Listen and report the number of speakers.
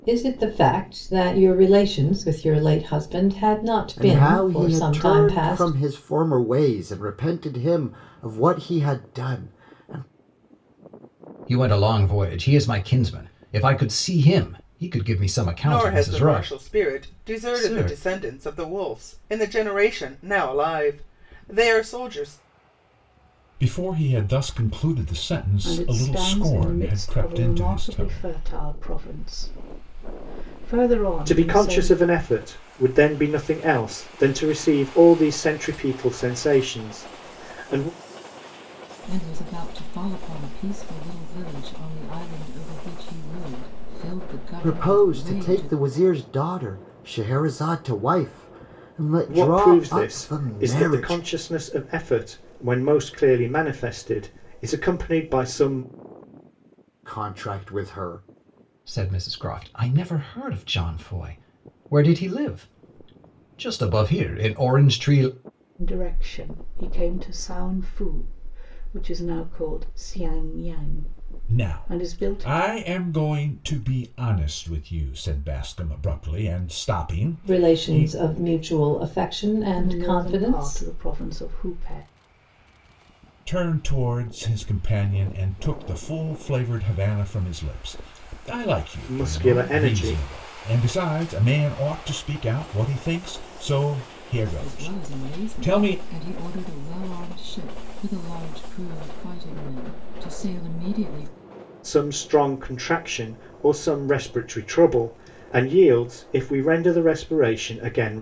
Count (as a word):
eight